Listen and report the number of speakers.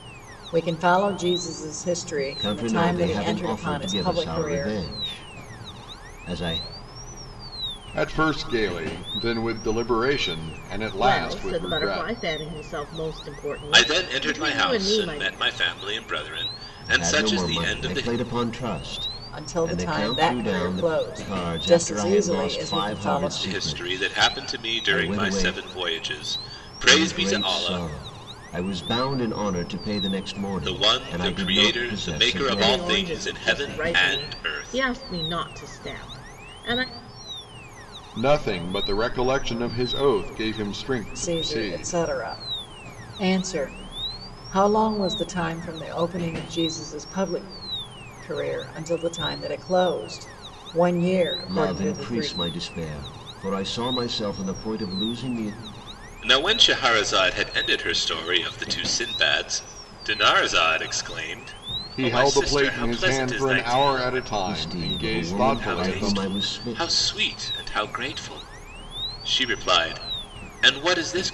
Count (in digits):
5